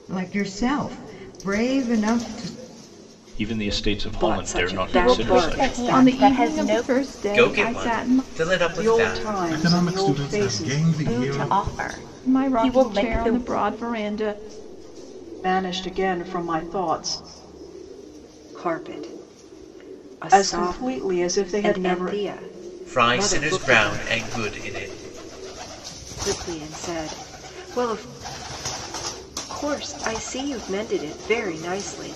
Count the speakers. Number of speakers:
8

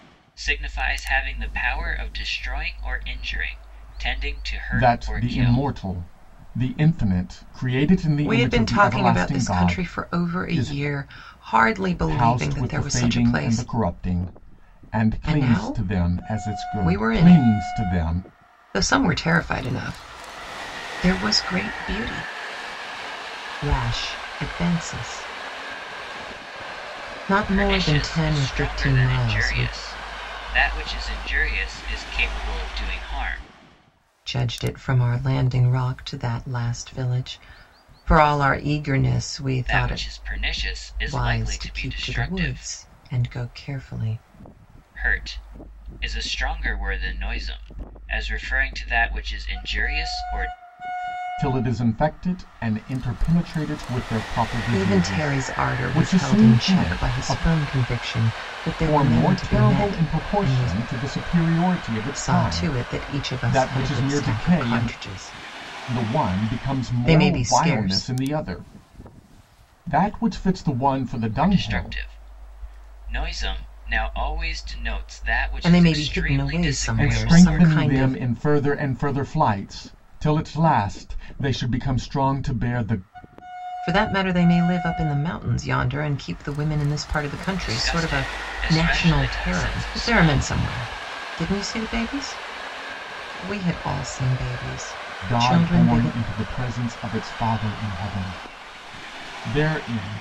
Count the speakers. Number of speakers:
3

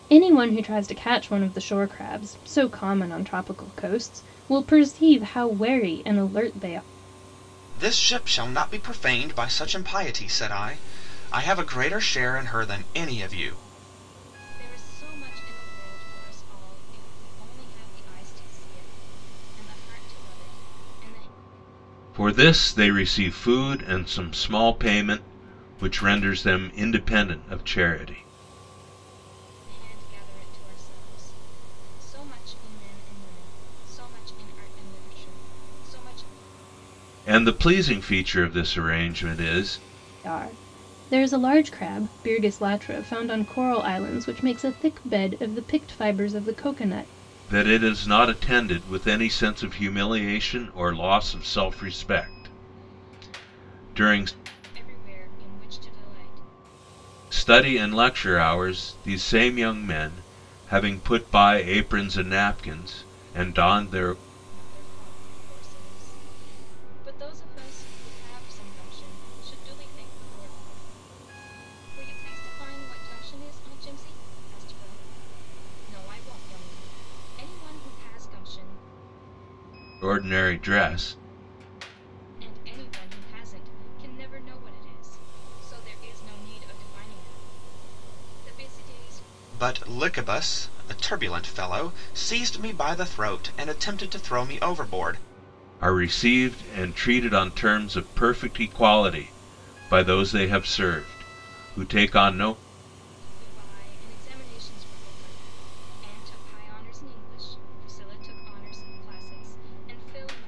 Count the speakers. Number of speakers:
4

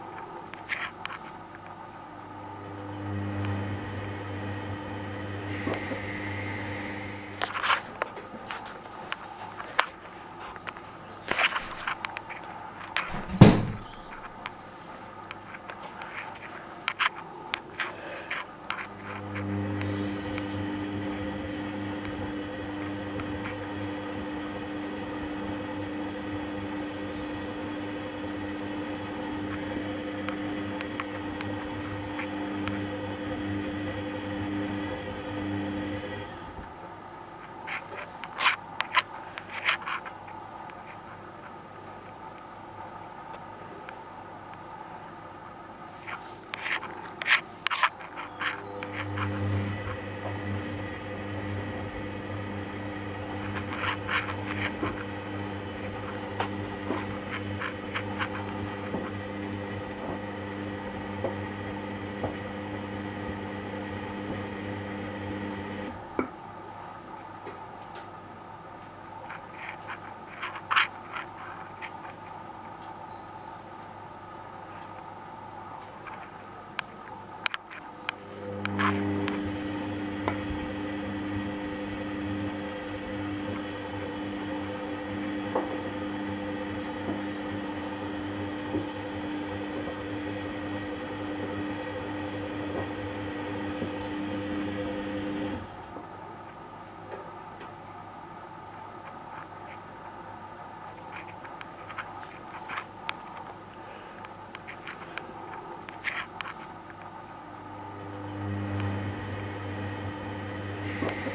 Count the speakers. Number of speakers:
0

